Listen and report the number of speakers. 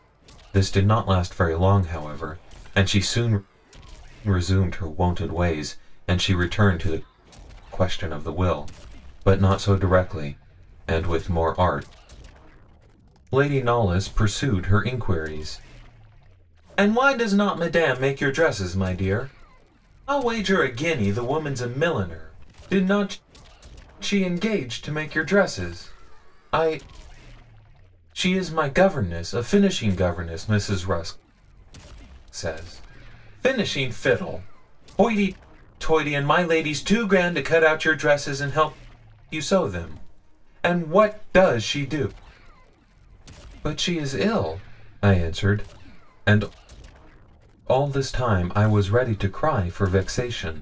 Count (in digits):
1